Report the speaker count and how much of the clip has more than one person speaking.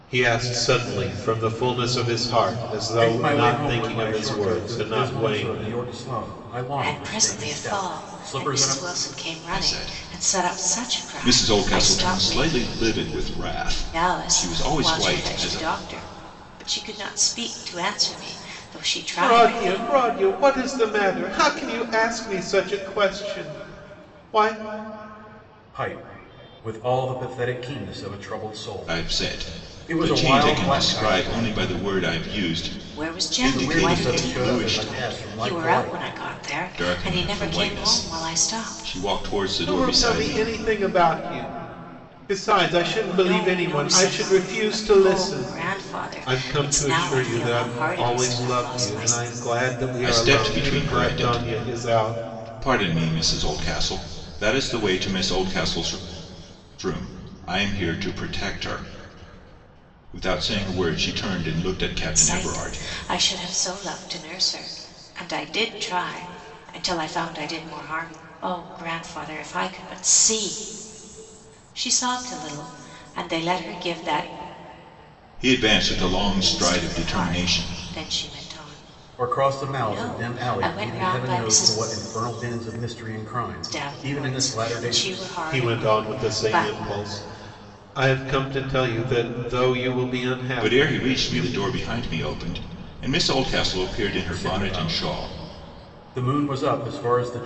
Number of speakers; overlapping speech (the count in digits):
4, about 37%